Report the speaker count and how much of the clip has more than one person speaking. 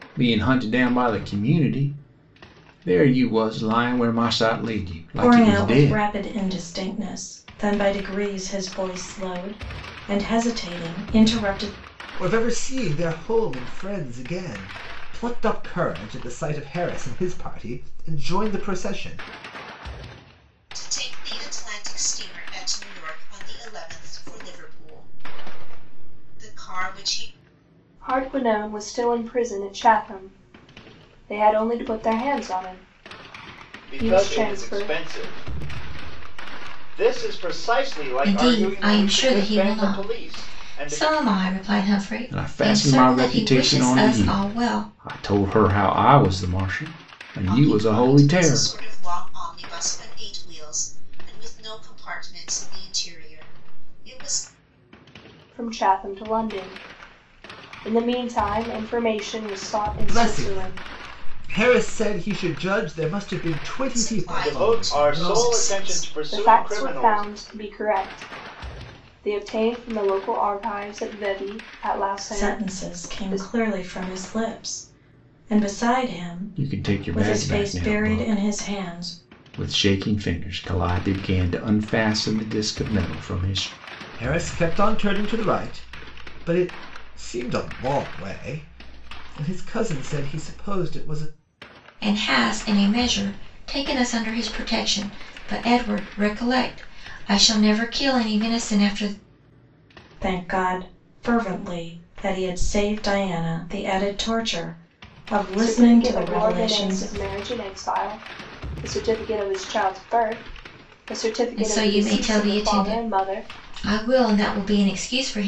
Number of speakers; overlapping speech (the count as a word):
seven, about 18%